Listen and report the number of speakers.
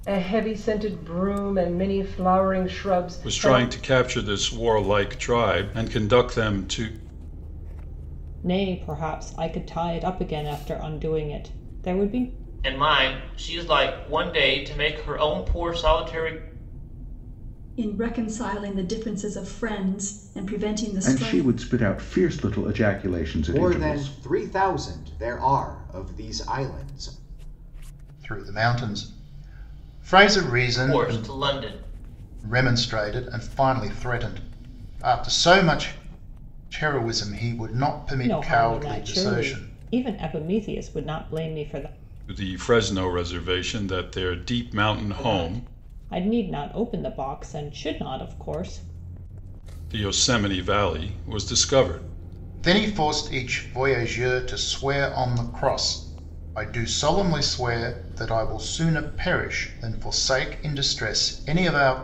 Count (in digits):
8